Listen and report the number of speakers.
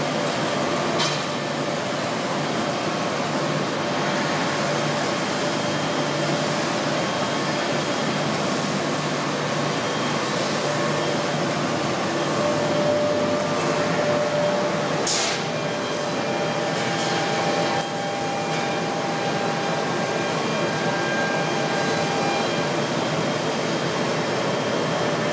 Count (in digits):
0